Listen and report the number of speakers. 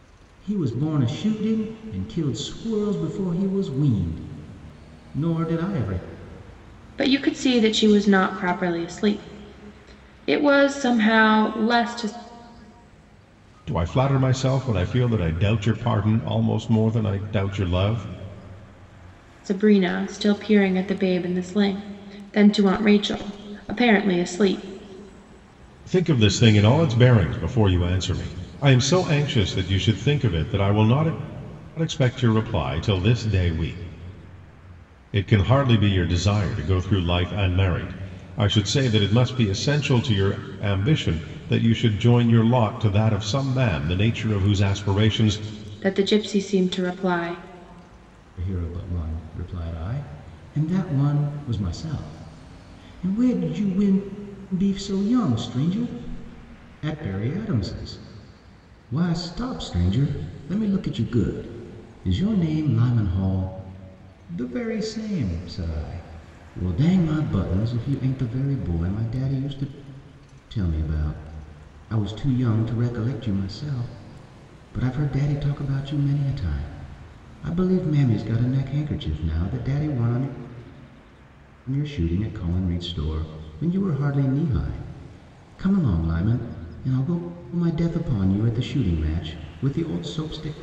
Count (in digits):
3